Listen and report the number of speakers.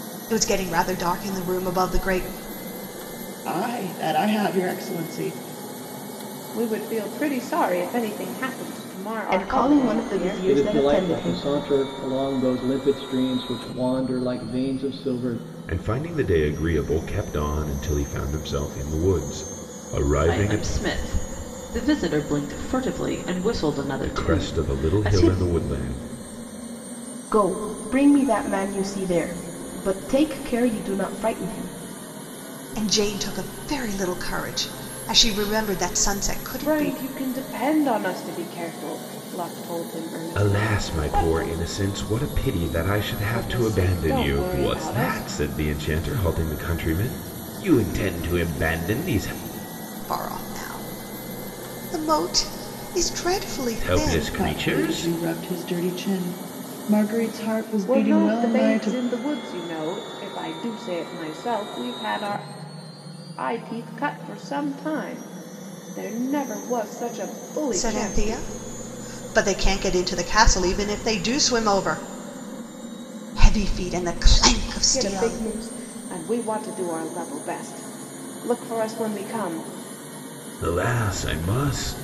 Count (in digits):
7